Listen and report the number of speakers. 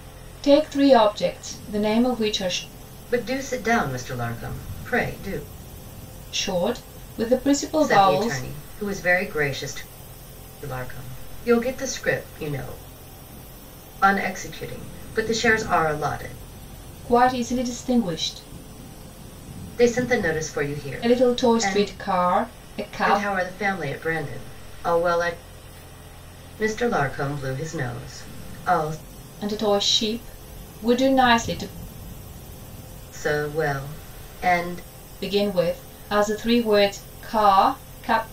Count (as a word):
two